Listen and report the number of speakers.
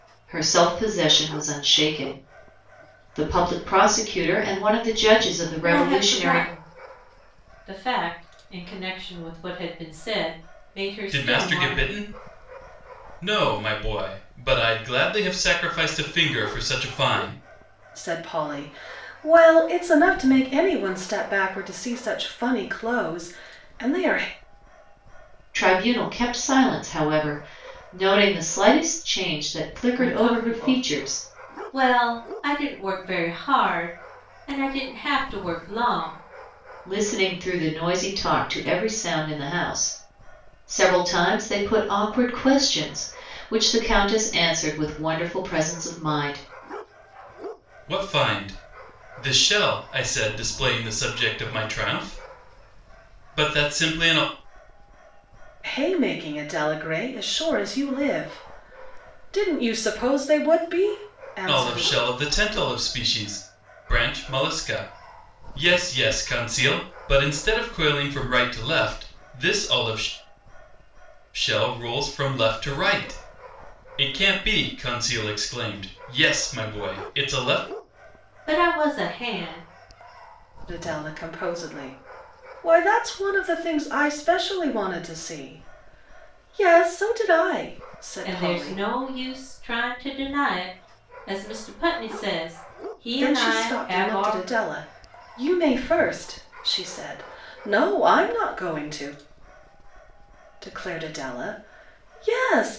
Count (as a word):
four